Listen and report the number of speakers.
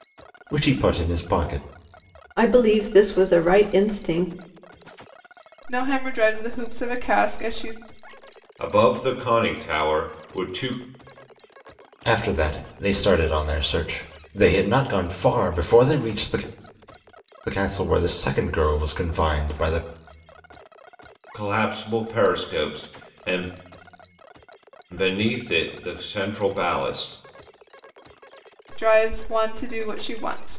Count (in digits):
4